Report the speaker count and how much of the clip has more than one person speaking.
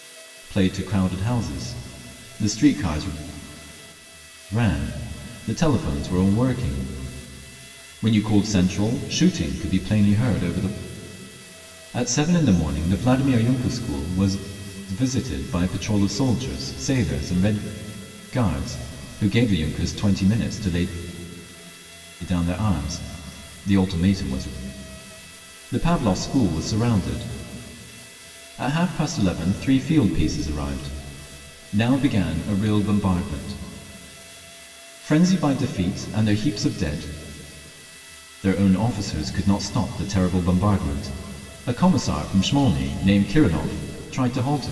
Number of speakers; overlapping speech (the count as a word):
one, no overlap